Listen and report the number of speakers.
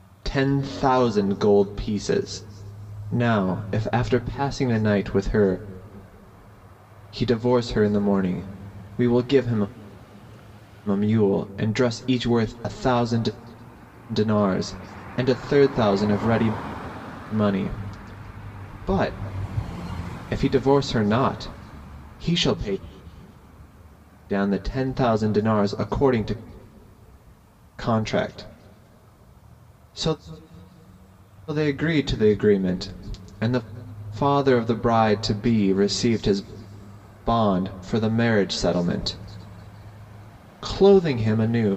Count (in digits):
1